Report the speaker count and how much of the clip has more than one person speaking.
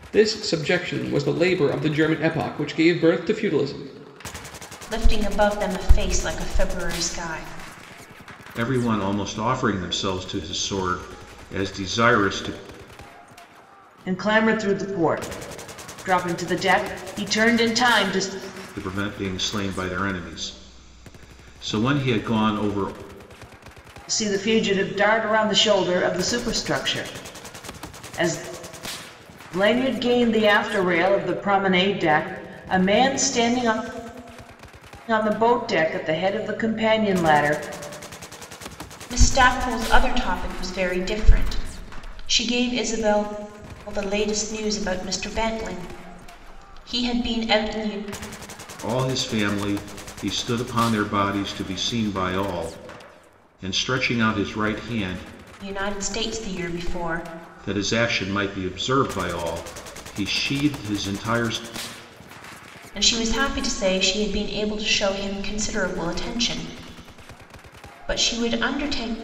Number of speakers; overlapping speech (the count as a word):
four, no overlap